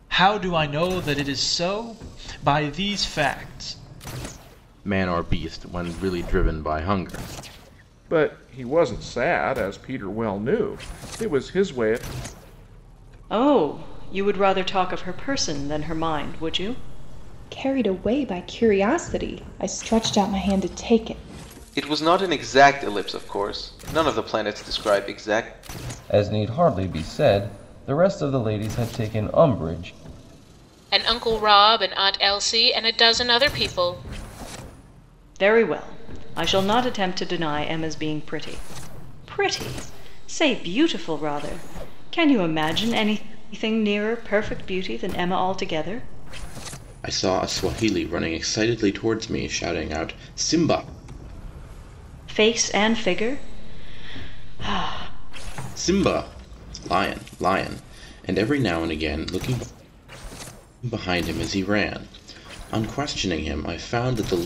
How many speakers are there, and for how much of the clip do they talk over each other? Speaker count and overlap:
8, no overlap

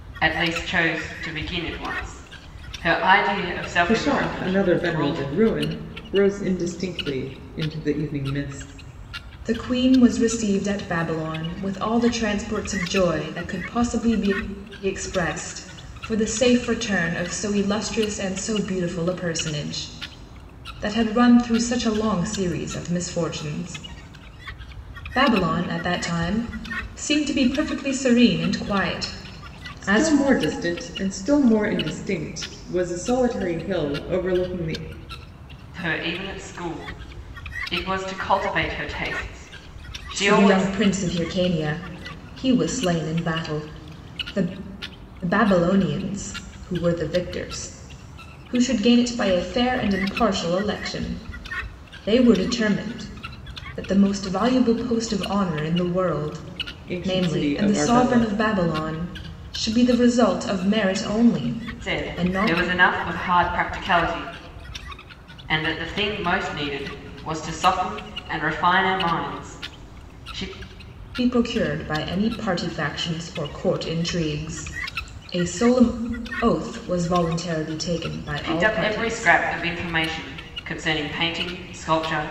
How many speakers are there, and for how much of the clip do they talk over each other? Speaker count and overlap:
3, about 7%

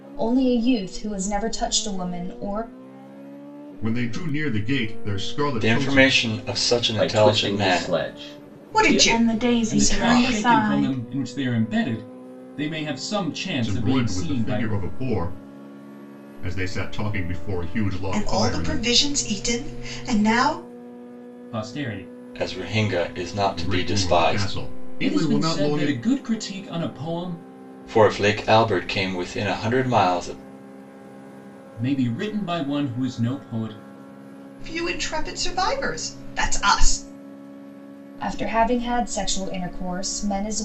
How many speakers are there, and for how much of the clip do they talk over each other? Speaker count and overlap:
7, about 19%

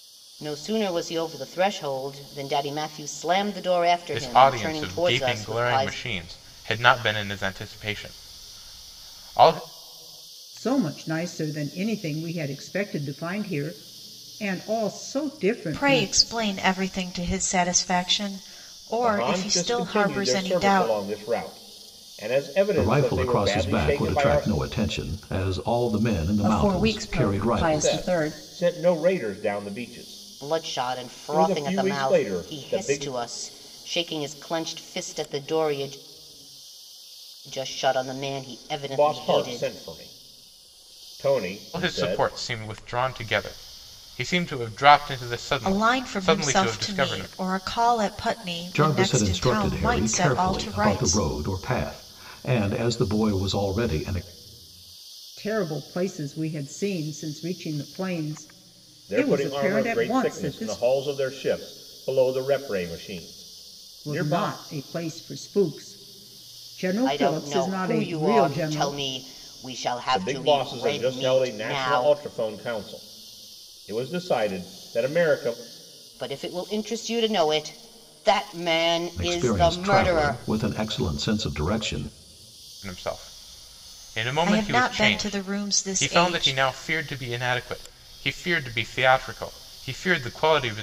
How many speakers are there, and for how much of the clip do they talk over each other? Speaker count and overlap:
7, about 29%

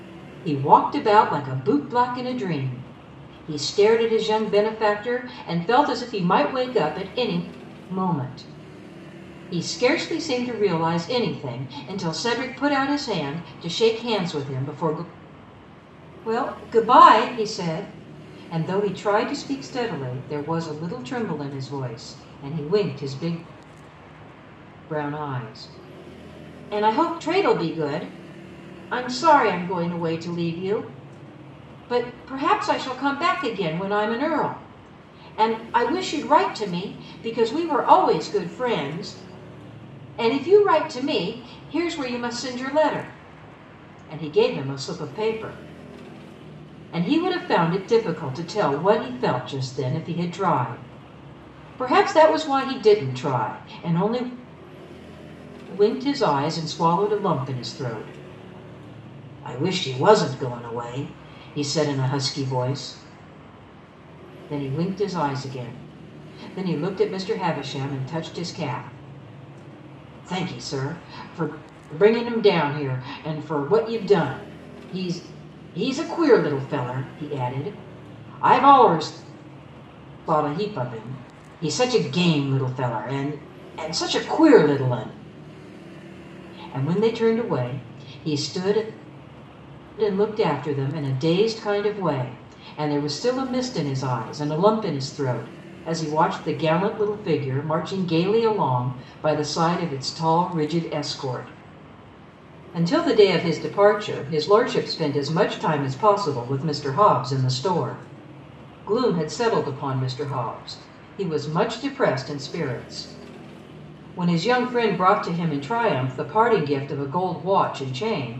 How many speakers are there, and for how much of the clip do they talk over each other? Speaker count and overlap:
1, no overlap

